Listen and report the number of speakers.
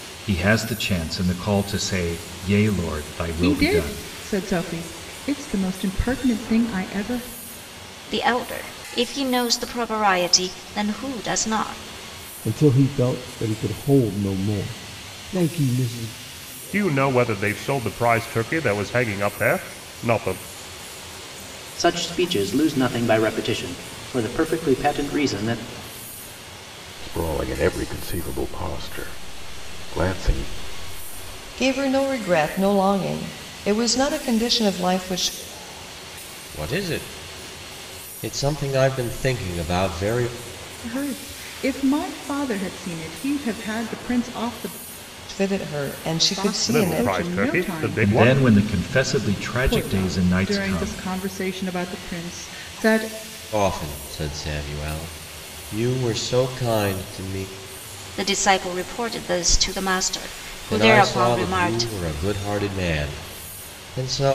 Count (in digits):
9